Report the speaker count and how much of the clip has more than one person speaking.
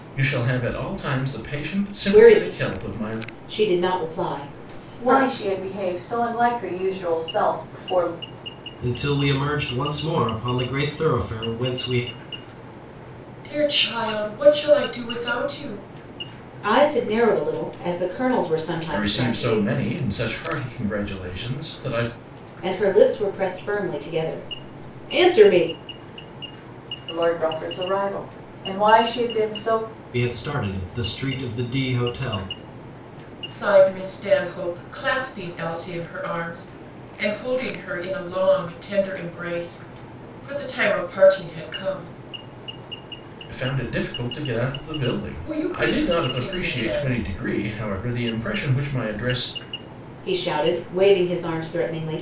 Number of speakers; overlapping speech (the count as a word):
five, about 8%